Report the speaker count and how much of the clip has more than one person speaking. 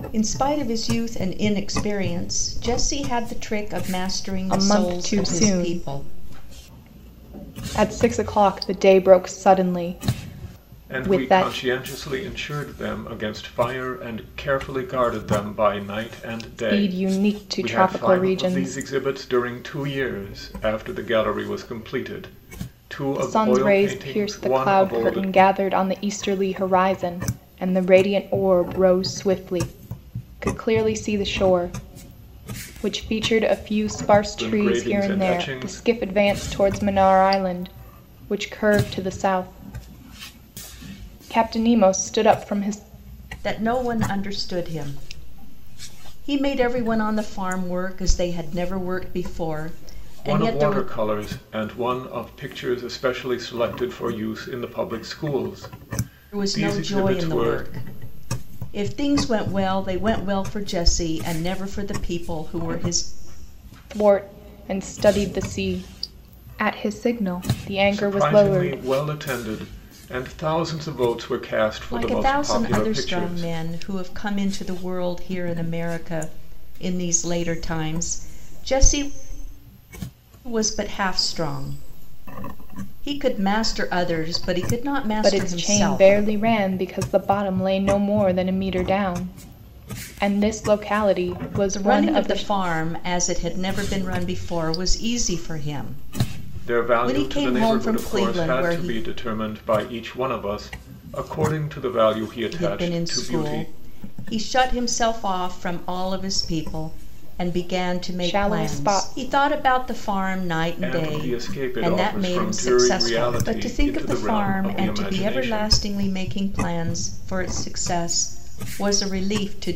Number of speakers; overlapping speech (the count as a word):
three, about 20%